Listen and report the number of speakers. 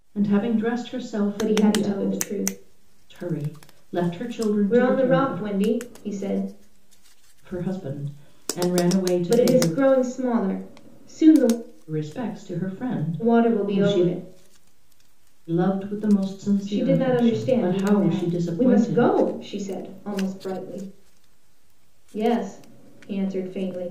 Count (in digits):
2